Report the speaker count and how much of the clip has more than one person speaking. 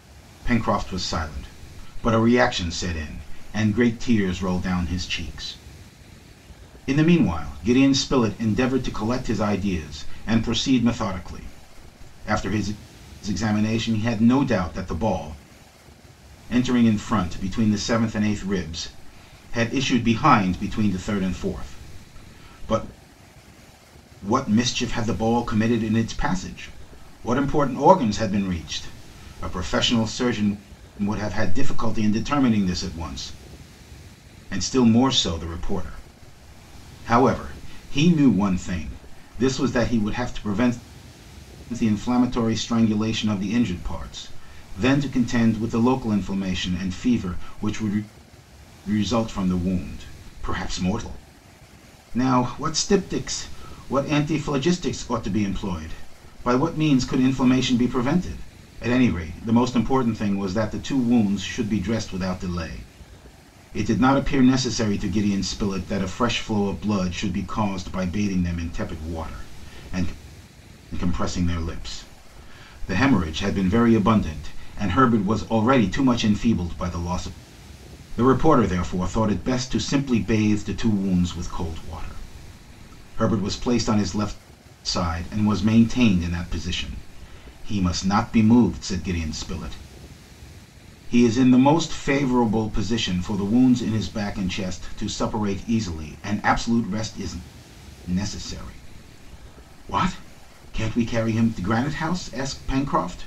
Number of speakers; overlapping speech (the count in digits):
1, no overlap